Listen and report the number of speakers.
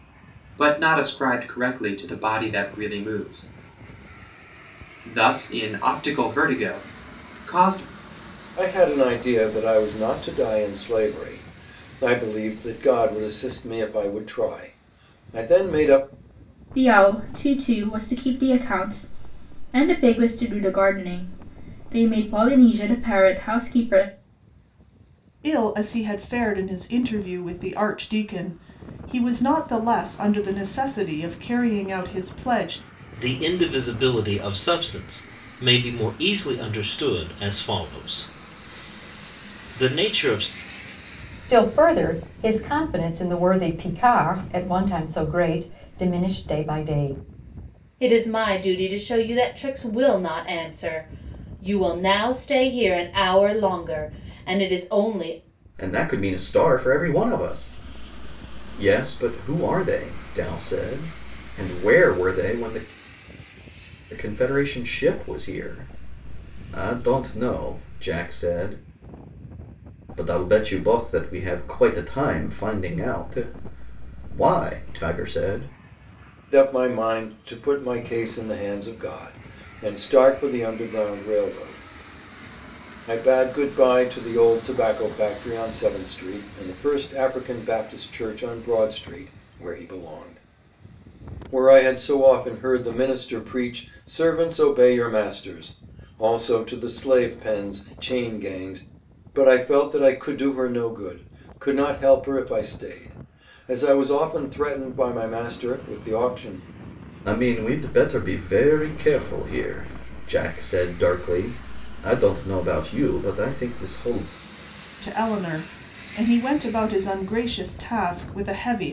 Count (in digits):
8